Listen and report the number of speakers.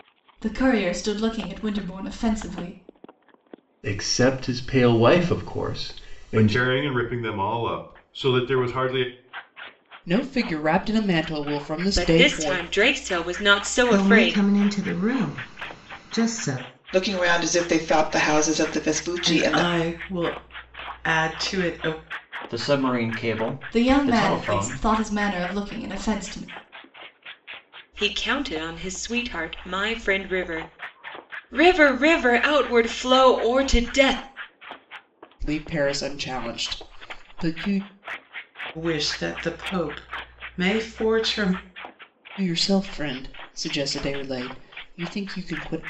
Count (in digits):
9